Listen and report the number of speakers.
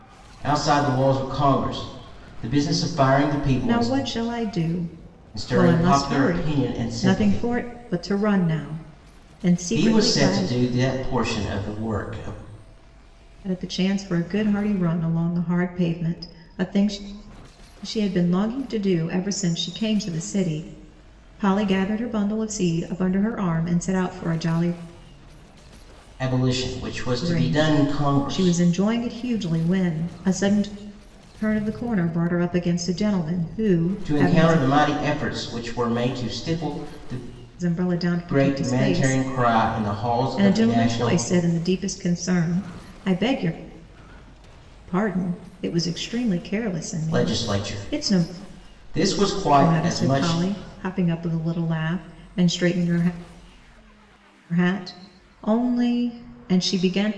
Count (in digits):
2